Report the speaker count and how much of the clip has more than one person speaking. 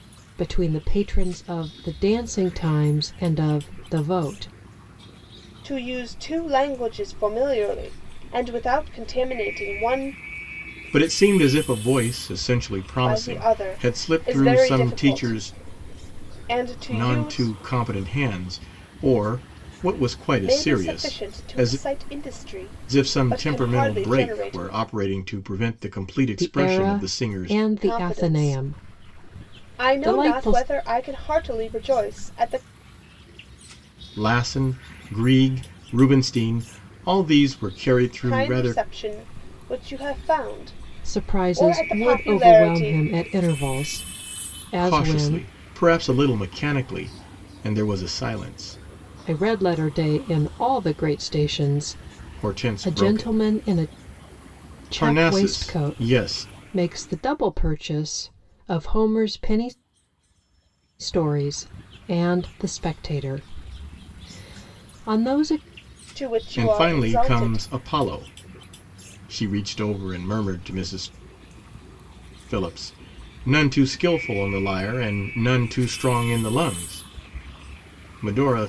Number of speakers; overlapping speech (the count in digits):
3, about 23%